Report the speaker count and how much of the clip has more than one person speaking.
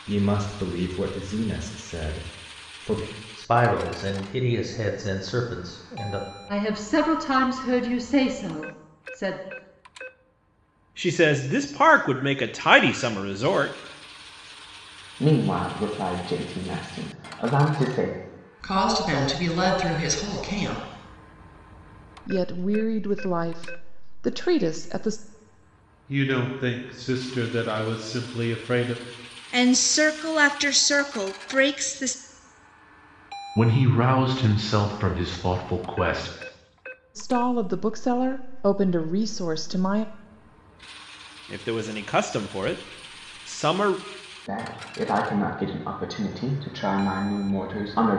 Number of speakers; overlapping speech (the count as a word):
ten, no overlap